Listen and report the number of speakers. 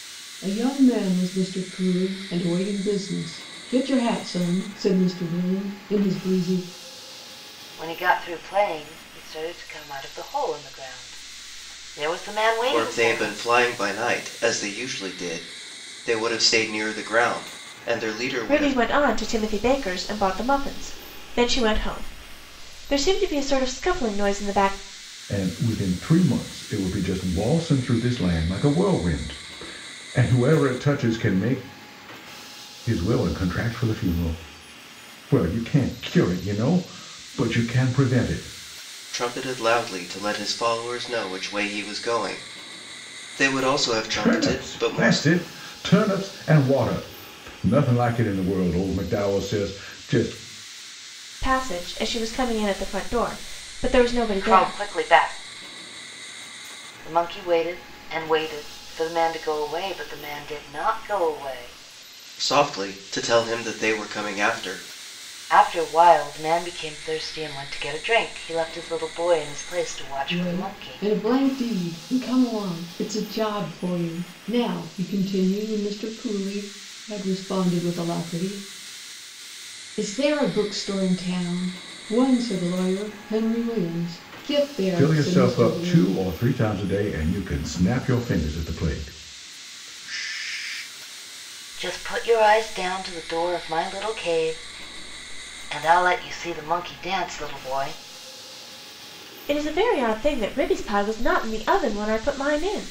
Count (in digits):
5